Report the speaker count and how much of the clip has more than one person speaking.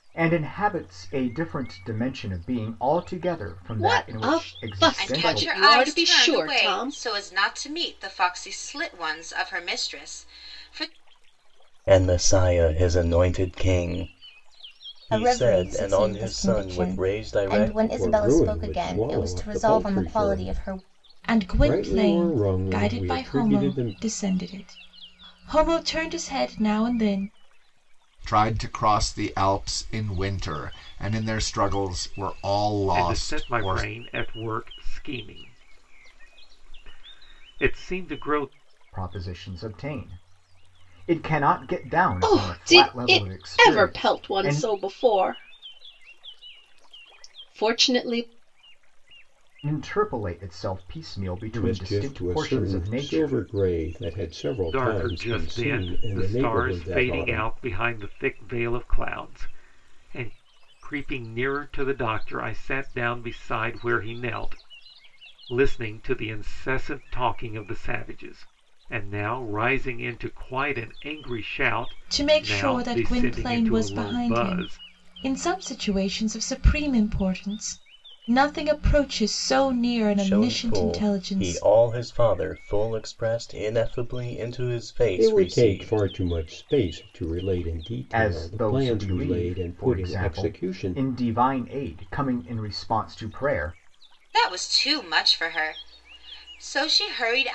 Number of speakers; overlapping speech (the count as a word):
nine, about 29%